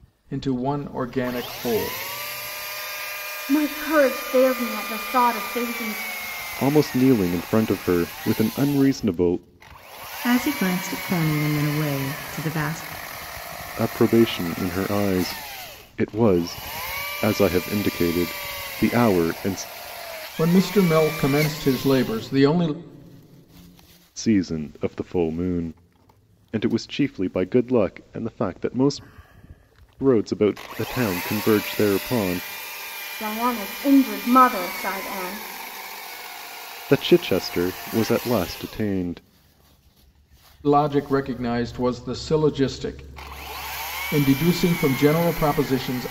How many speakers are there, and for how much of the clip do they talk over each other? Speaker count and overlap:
4, no overlap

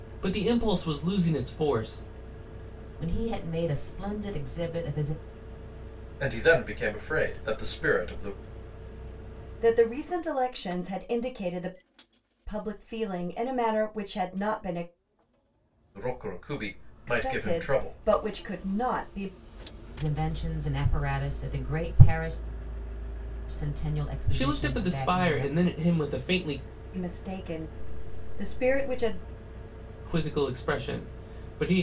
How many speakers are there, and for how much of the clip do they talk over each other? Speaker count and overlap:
4, about 7%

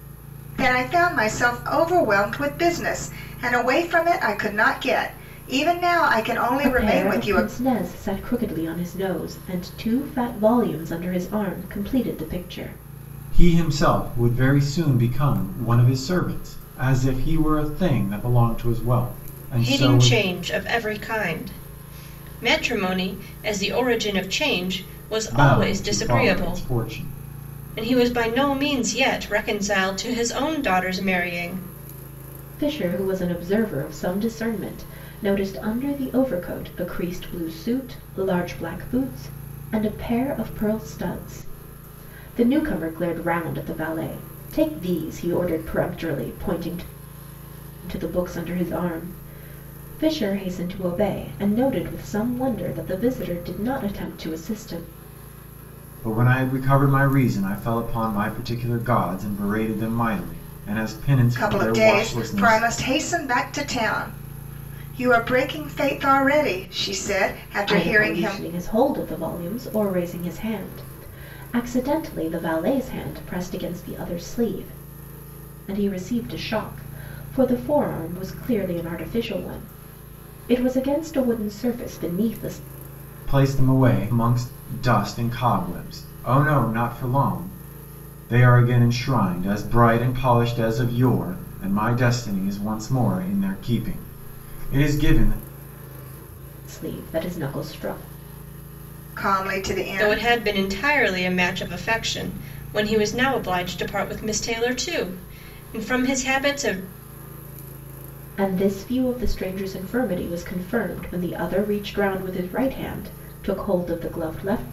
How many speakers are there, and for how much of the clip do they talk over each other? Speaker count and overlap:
4, about 5%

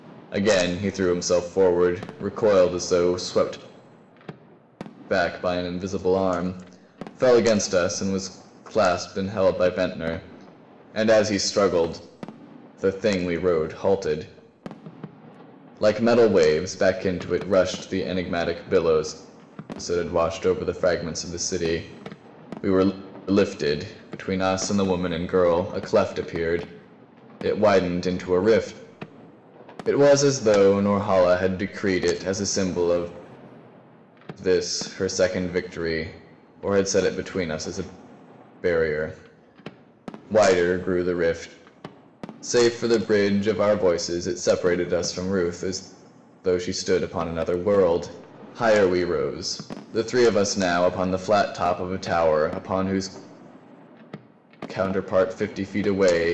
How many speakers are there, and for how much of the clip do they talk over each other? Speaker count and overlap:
1, no overlap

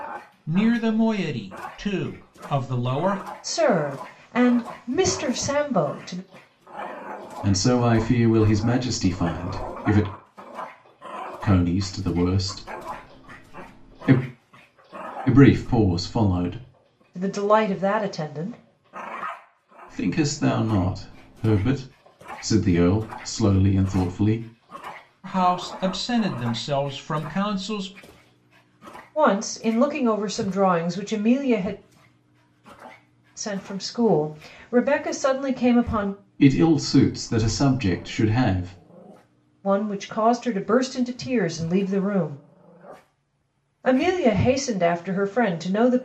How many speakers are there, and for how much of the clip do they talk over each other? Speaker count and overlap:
3, no overlap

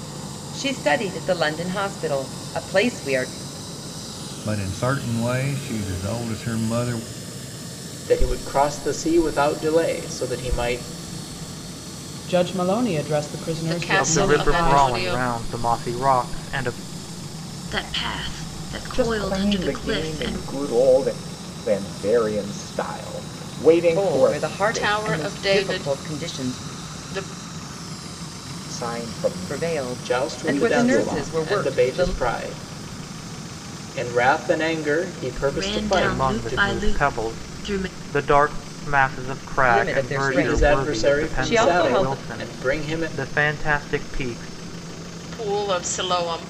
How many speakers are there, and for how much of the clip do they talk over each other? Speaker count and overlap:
8, about 31%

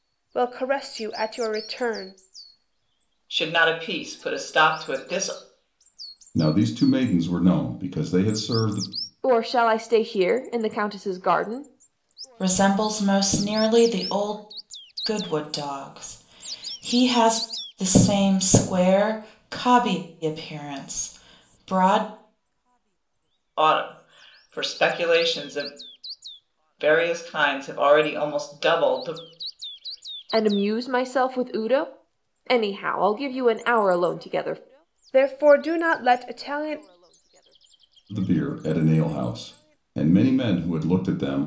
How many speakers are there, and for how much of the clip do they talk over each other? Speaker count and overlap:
5, no overlap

